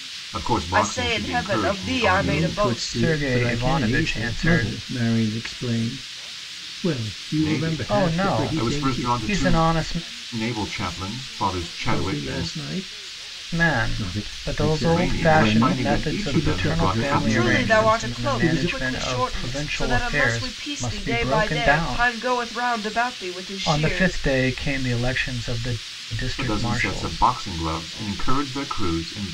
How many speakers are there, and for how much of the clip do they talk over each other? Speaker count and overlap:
4, about 56%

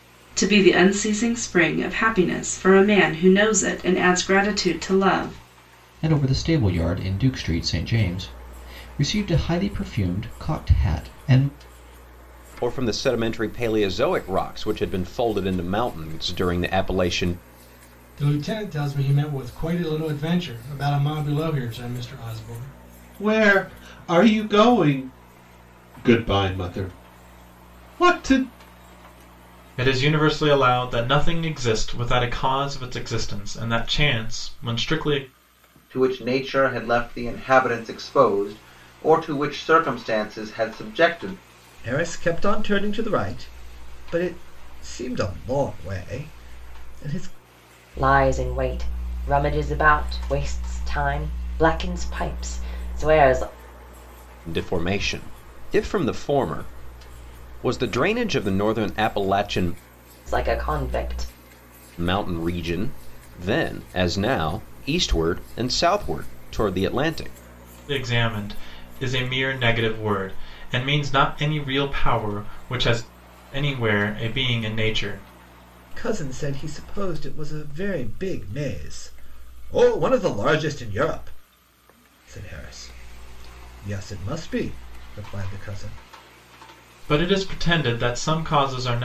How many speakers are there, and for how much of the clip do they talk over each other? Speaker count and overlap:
9, no overlap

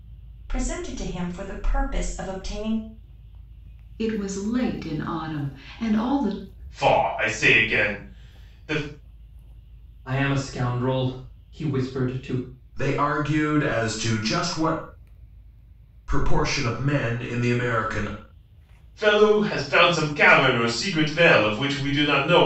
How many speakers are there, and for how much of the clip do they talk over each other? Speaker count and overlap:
5, no overlap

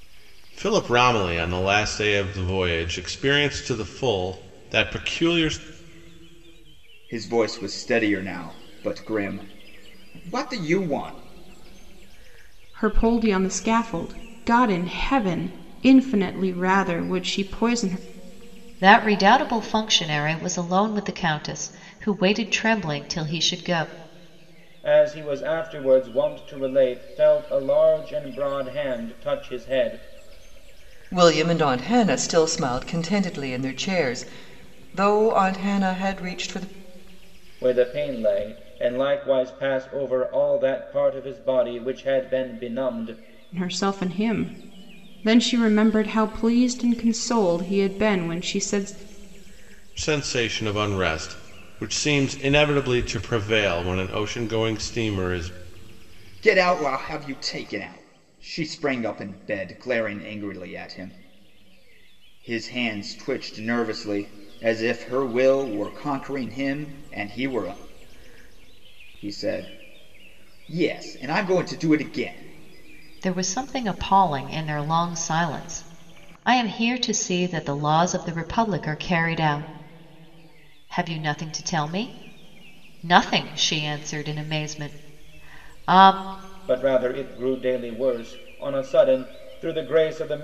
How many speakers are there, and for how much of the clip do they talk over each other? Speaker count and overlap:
6, no overlap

